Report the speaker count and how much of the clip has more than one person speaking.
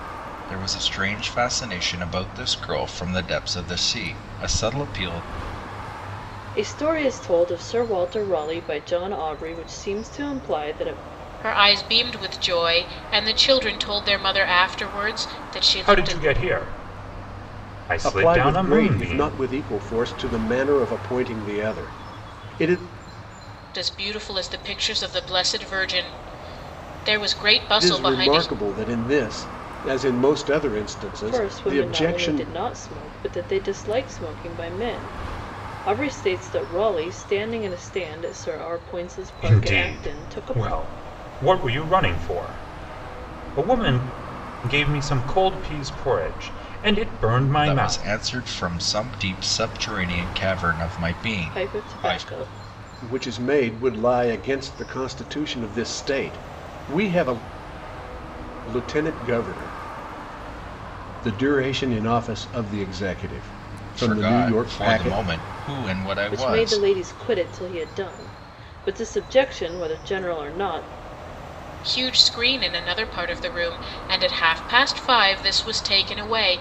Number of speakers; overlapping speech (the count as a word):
five, about 11%